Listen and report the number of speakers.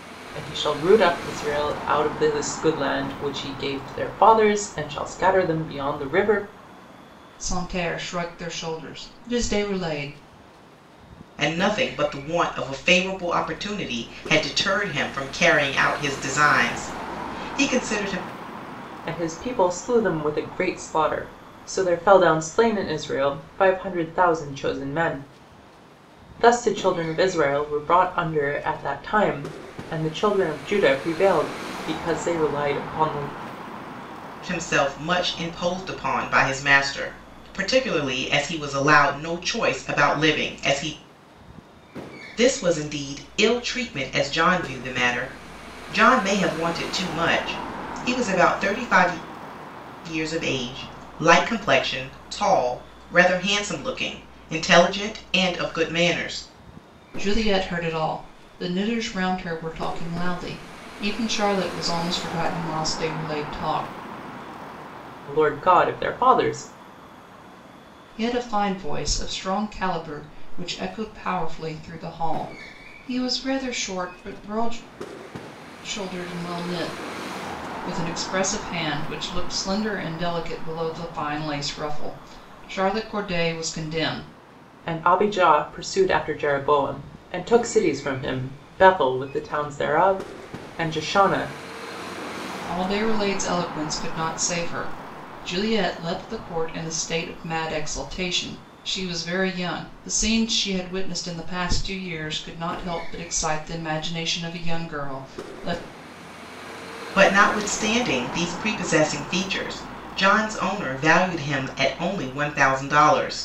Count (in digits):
3